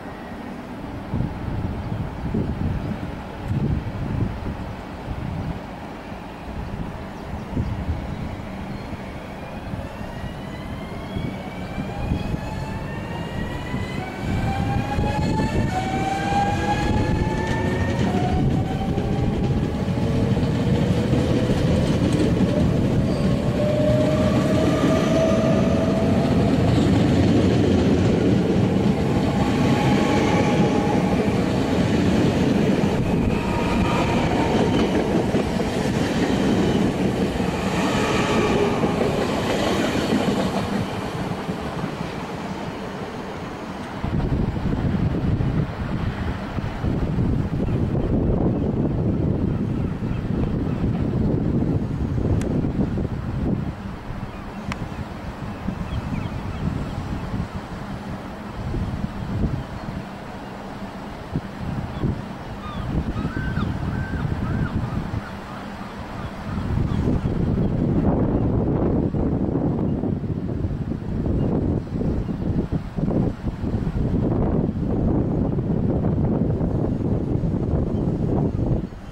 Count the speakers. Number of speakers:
0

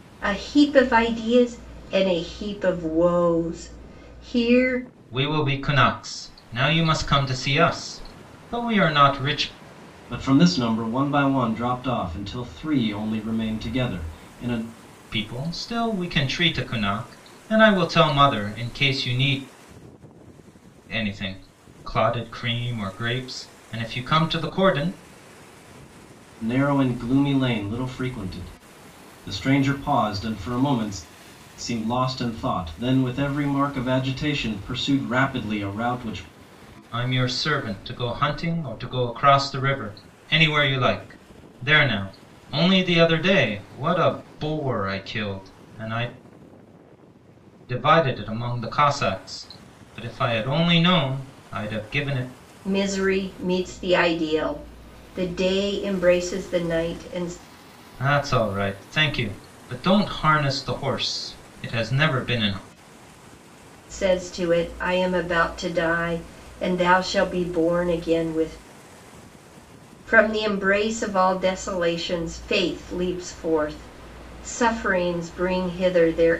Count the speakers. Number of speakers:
3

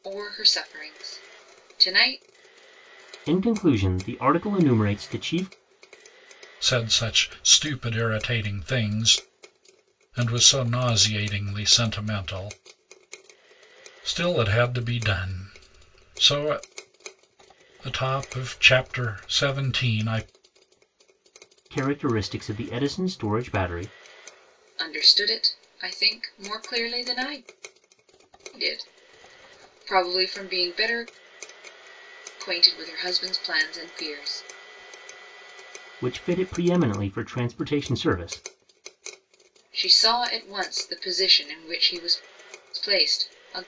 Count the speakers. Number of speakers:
3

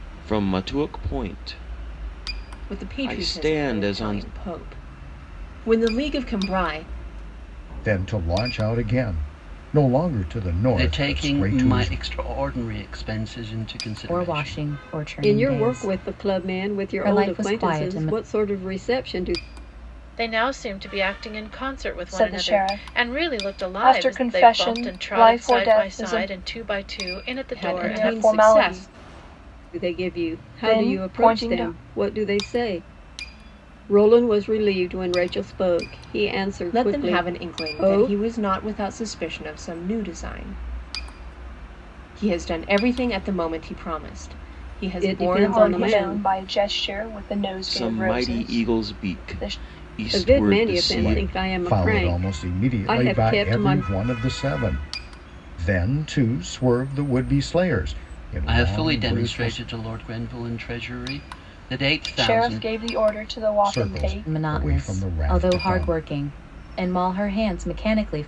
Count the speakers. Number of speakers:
8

